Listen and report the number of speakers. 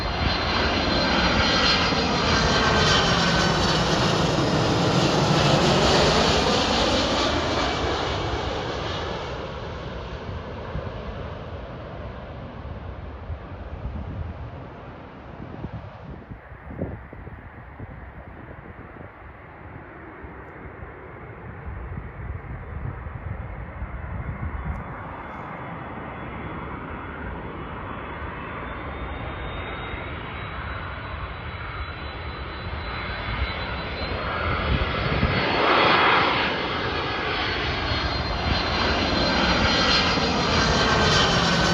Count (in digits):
0